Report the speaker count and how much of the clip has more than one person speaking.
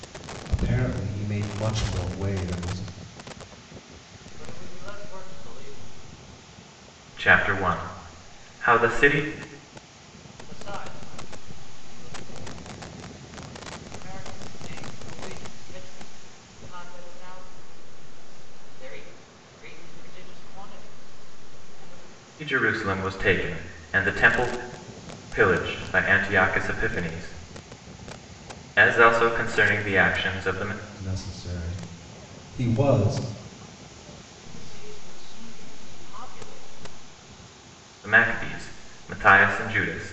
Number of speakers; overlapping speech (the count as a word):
three, no overlap